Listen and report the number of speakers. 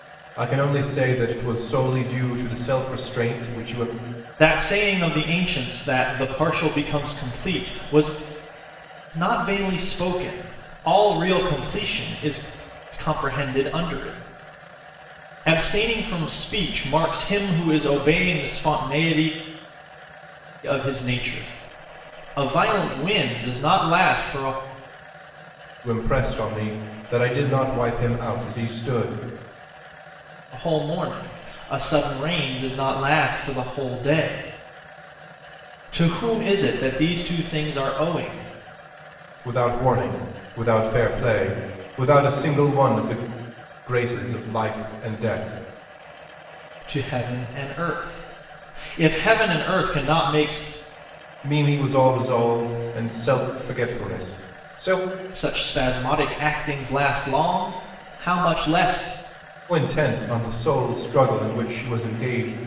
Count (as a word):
two